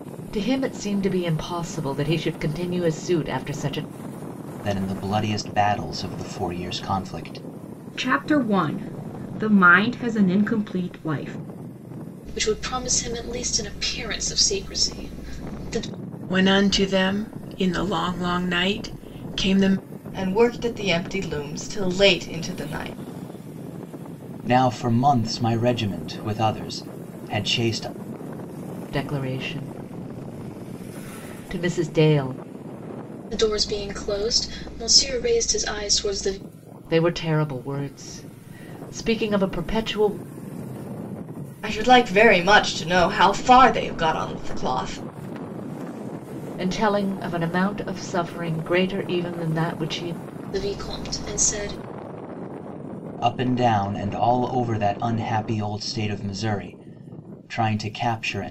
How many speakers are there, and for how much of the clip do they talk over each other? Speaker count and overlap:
6, no overlap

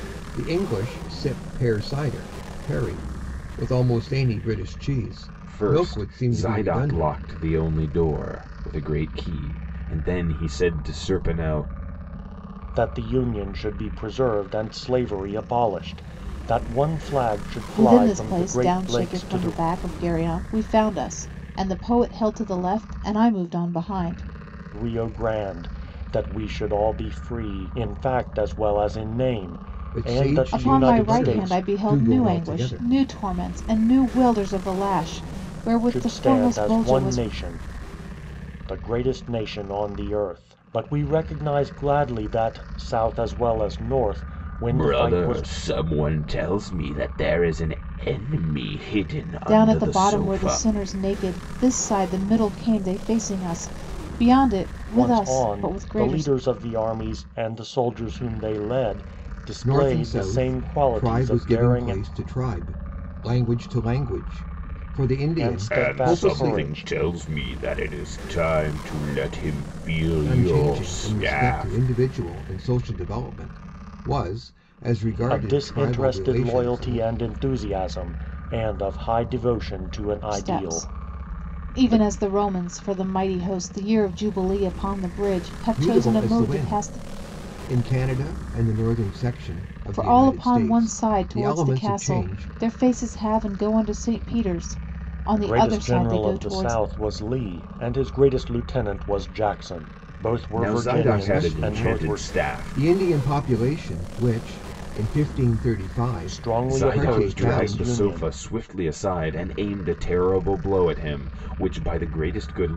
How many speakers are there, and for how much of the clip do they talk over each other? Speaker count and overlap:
4, about 27%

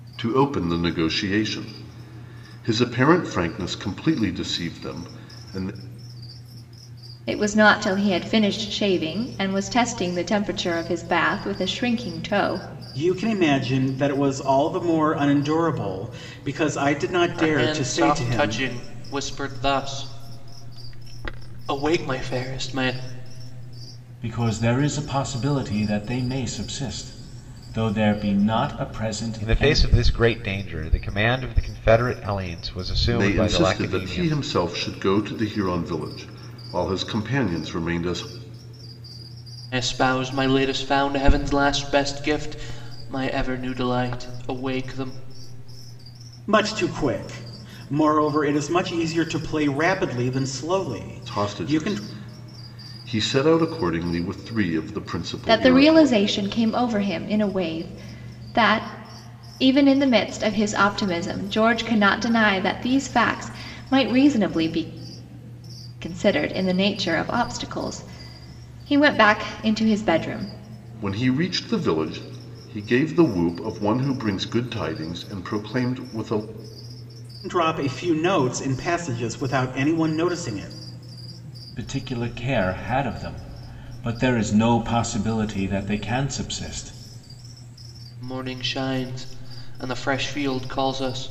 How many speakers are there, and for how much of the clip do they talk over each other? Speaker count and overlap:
6, about 5%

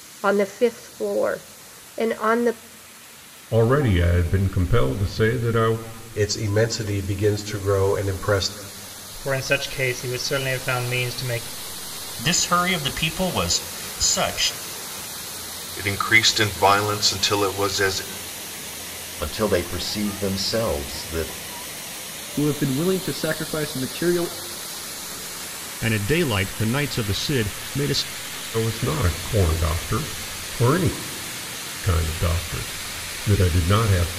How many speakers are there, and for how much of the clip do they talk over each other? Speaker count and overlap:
9, no overlap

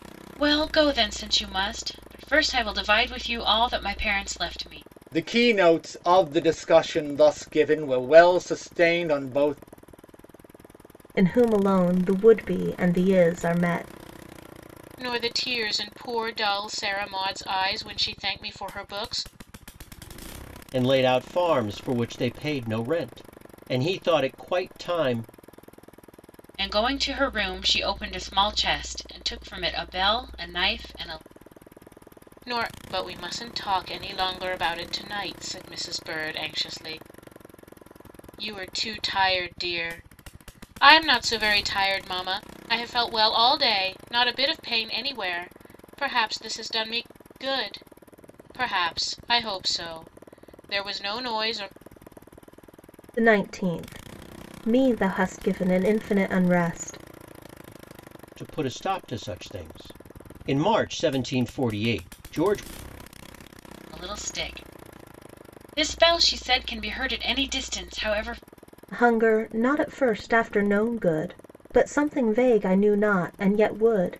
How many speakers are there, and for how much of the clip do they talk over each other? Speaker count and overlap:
5, no overlap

